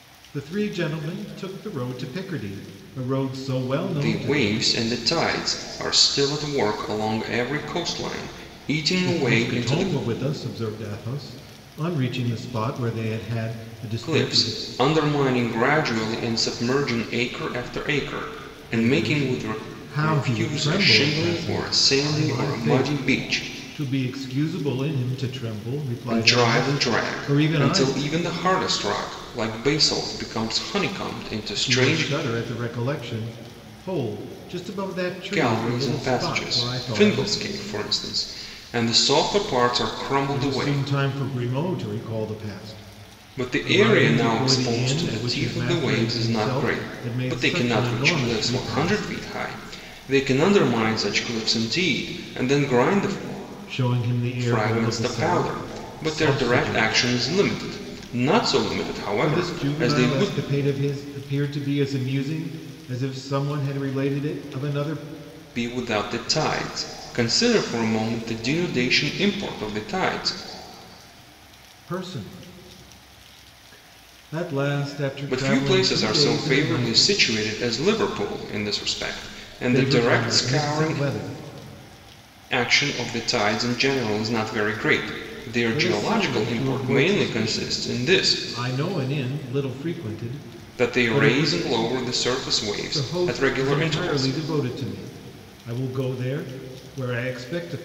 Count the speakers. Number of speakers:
two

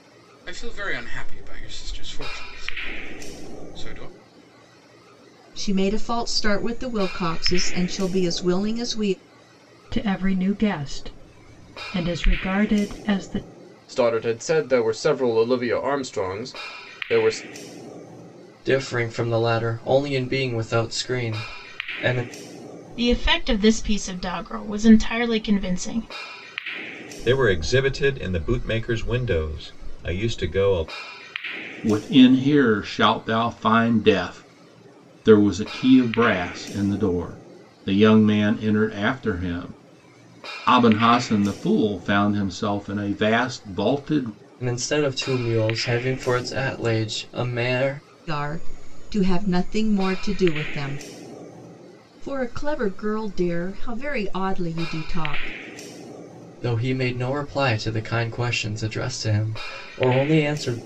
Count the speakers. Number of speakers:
eight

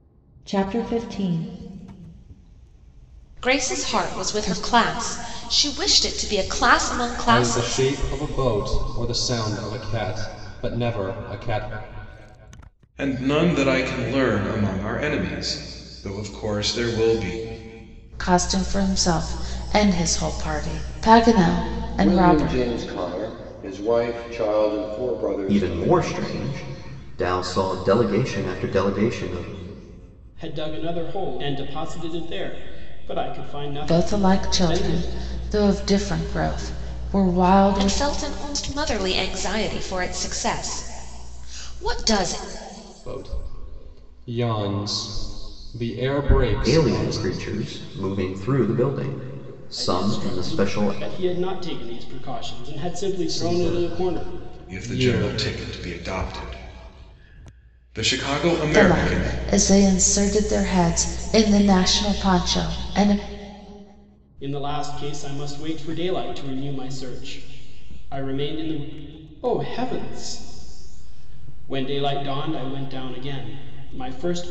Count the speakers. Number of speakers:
eight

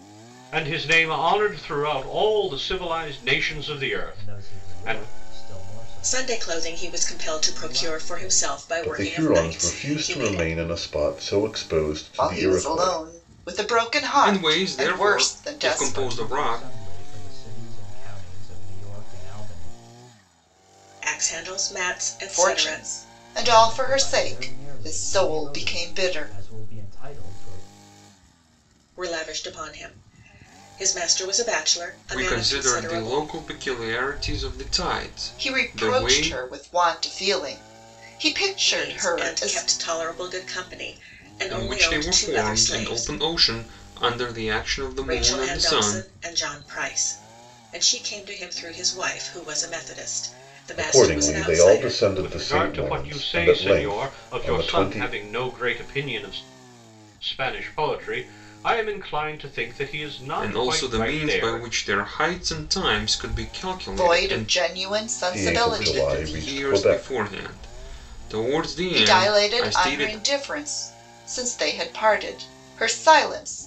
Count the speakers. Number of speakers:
six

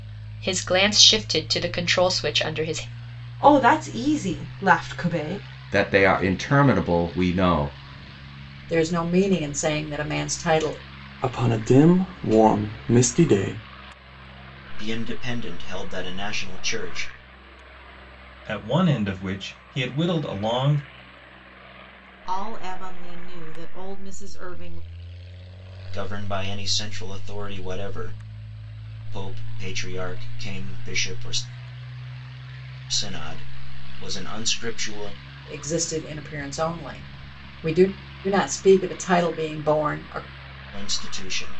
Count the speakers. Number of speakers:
eight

